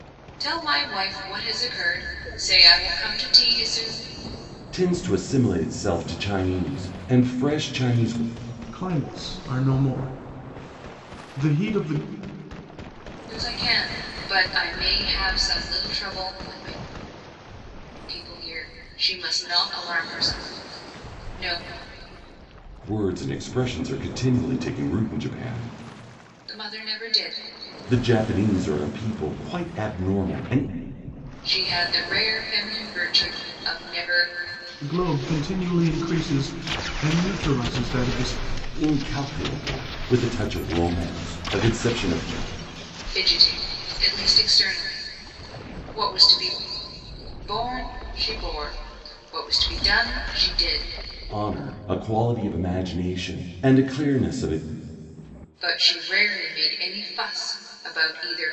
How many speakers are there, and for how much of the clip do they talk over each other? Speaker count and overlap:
3, no overlap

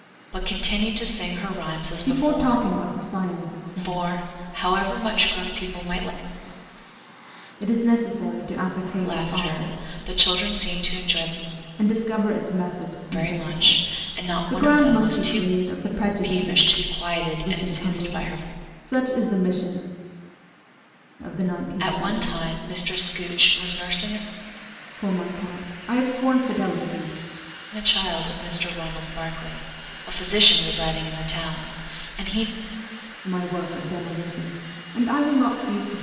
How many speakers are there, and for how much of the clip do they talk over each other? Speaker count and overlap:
2, about 17%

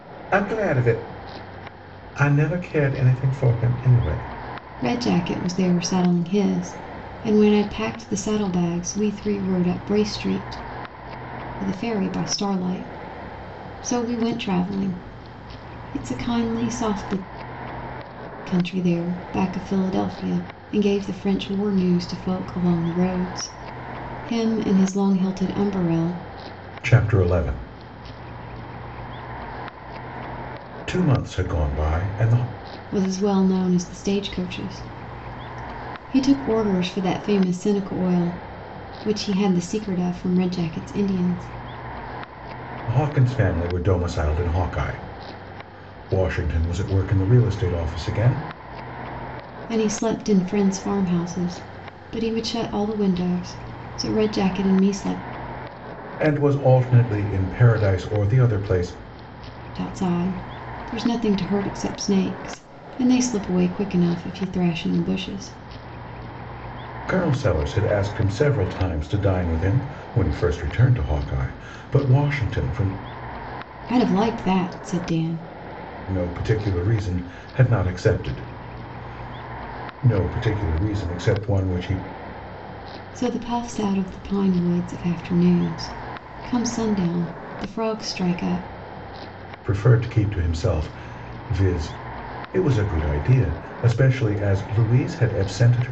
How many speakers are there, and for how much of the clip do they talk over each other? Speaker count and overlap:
2, no overlap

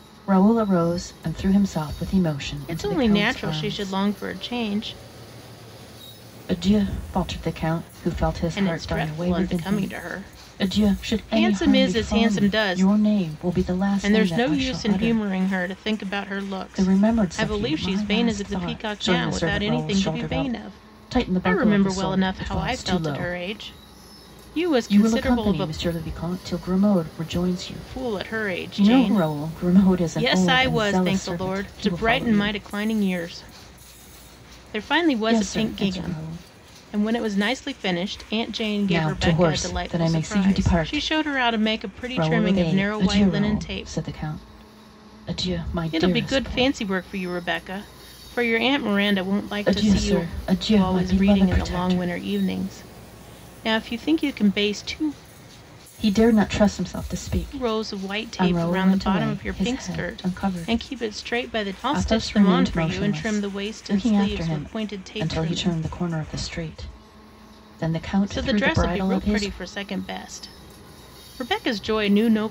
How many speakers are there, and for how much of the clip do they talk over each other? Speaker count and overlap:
2, about 51%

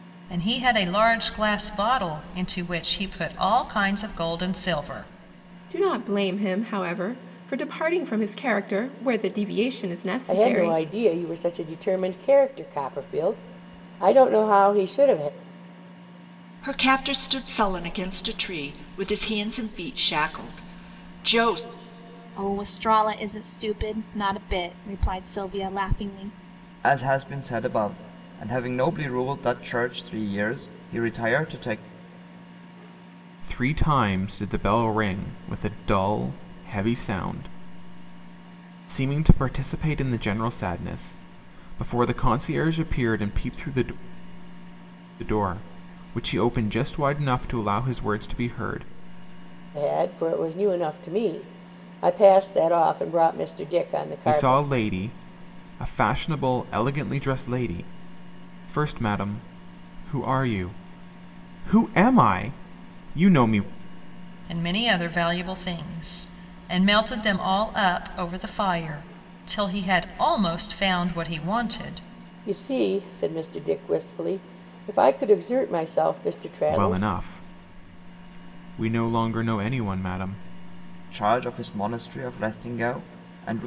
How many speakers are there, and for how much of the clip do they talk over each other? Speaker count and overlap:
7, about 2%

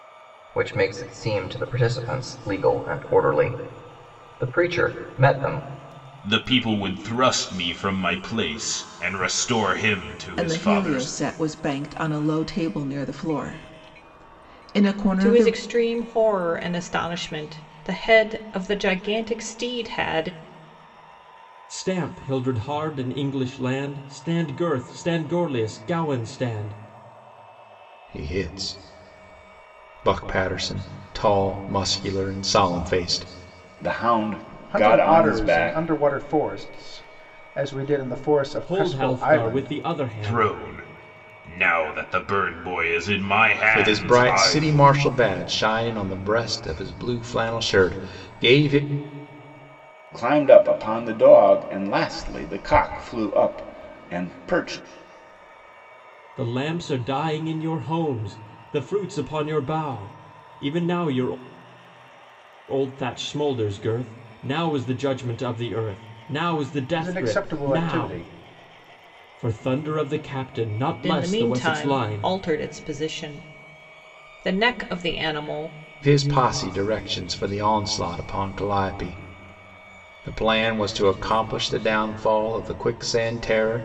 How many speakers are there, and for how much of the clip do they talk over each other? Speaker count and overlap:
8, about 9%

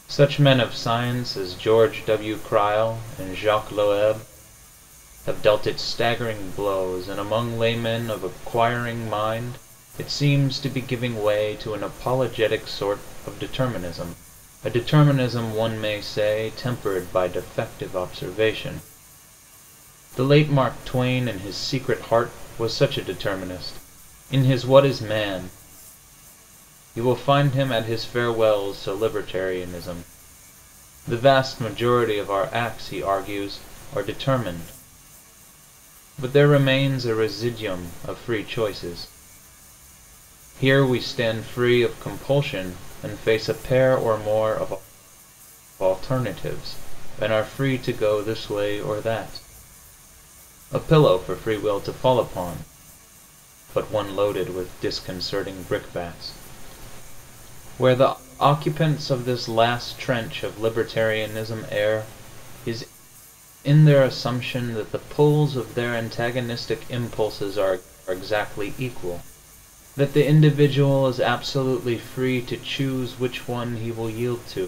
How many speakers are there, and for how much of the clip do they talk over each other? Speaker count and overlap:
1, no overlap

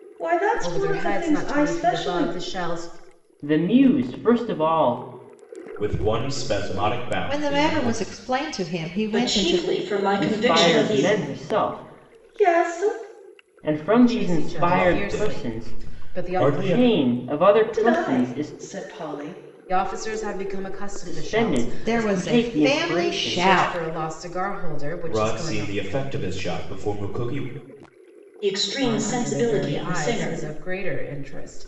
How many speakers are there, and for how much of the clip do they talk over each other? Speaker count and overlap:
6, about 43%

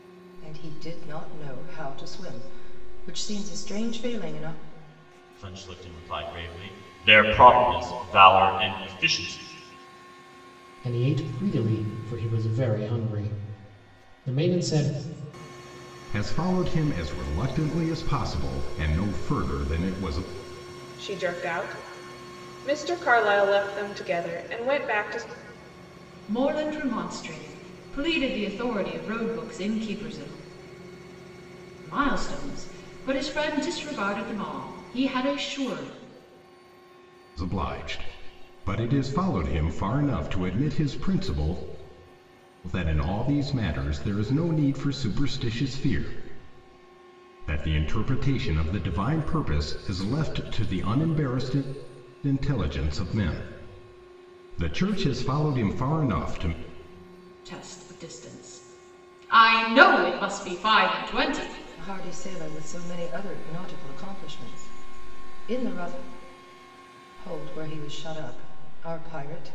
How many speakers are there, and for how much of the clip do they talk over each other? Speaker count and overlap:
6, no overlap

